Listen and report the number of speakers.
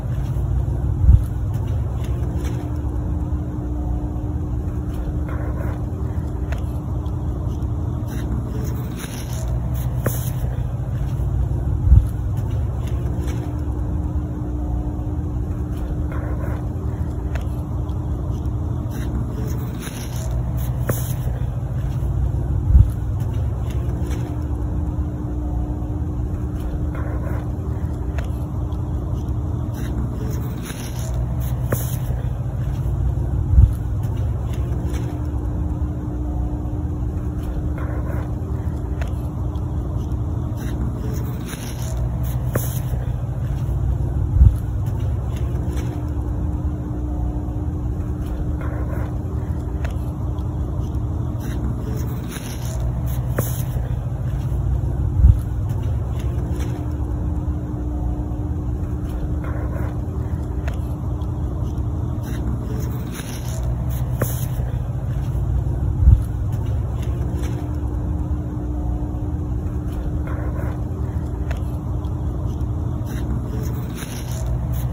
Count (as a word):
zero